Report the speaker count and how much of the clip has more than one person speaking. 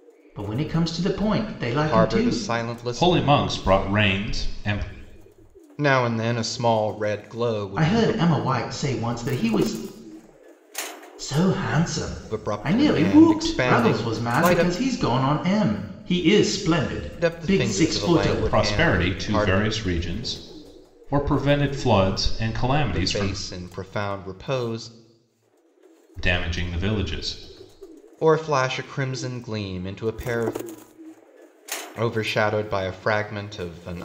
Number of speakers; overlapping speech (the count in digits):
3, about 20%